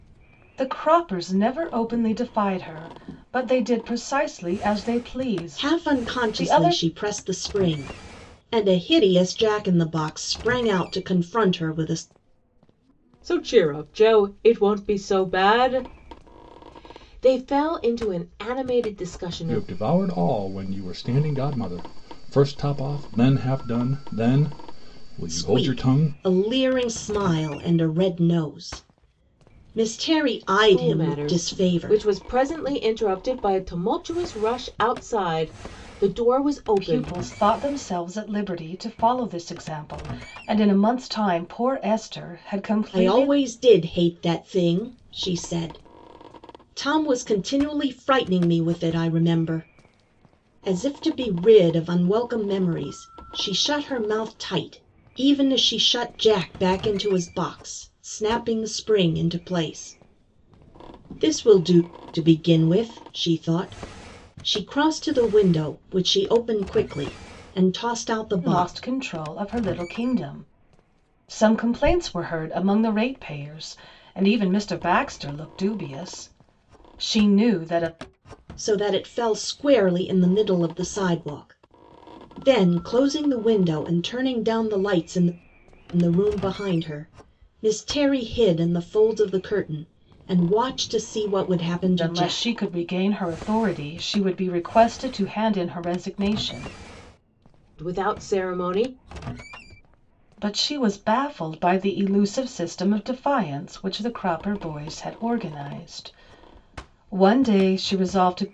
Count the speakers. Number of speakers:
4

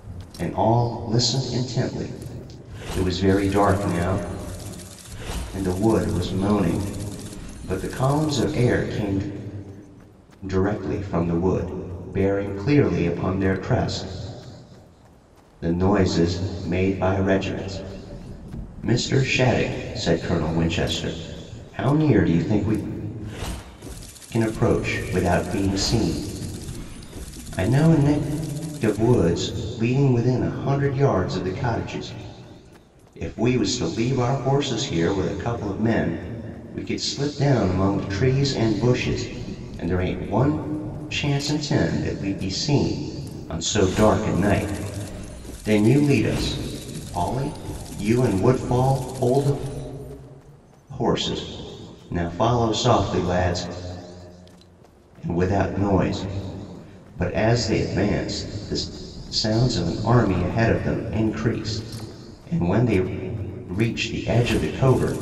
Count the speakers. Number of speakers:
1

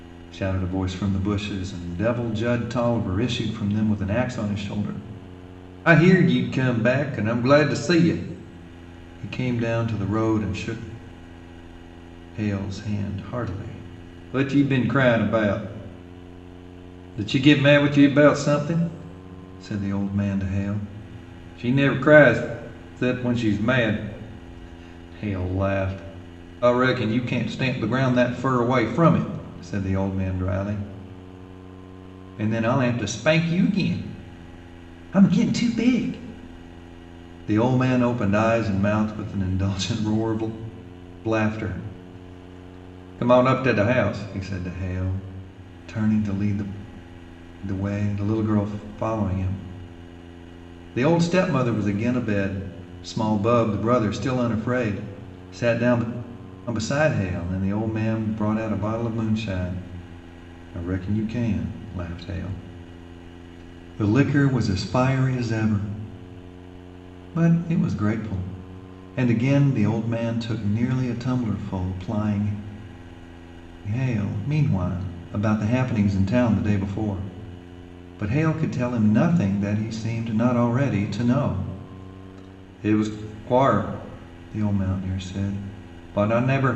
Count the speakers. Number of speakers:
1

